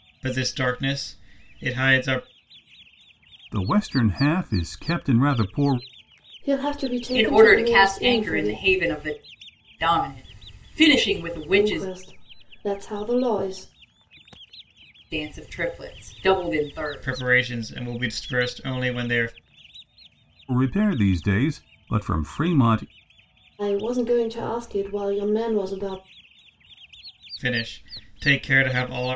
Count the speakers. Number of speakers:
4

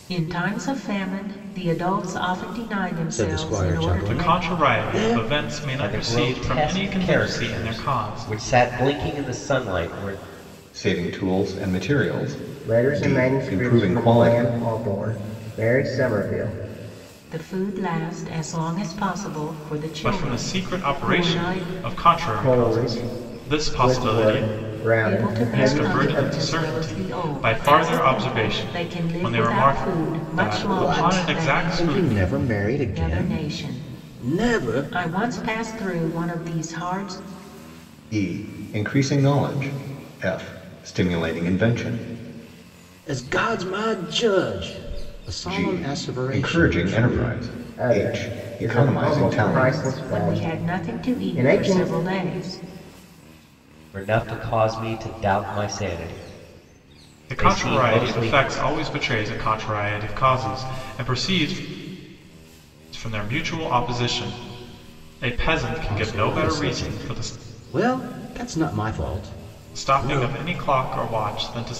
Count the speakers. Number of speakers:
6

